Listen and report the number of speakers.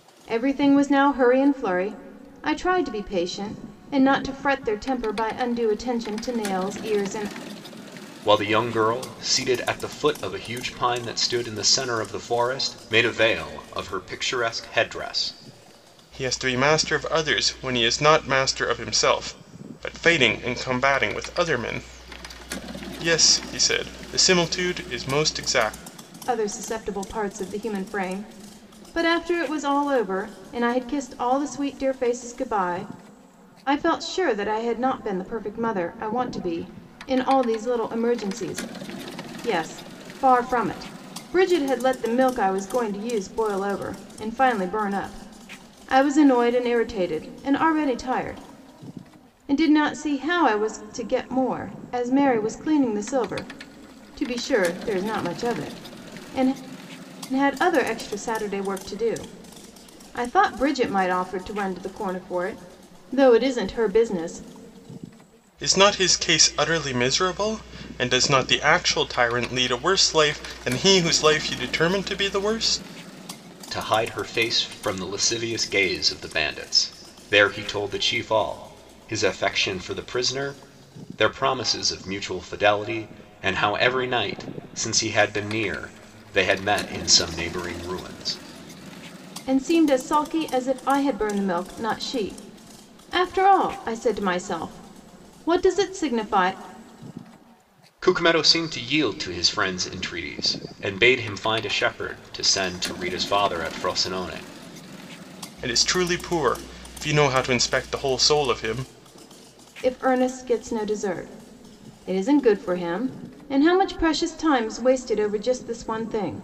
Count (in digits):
3